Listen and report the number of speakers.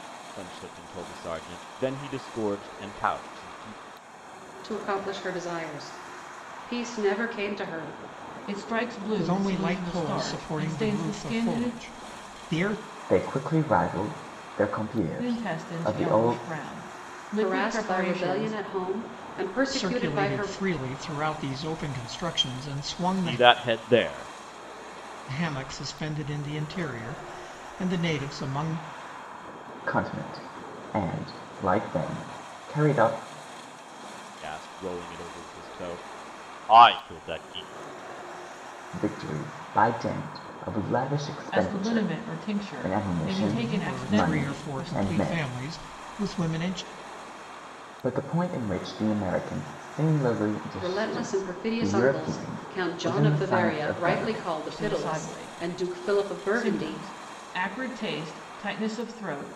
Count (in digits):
5